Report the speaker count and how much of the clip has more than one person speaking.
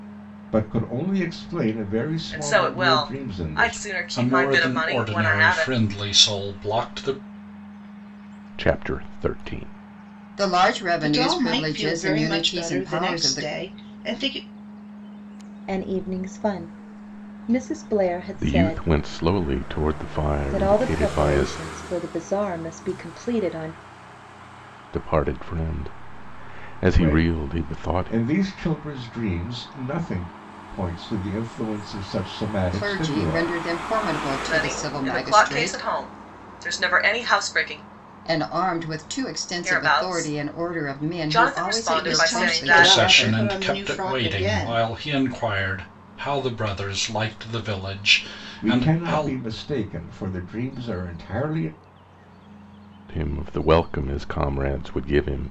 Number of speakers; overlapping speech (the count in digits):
7, about 30%